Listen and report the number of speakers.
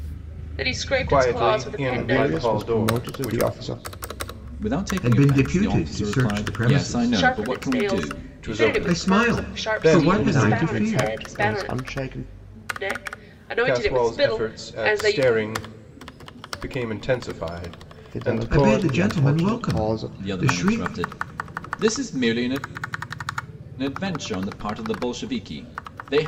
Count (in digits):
5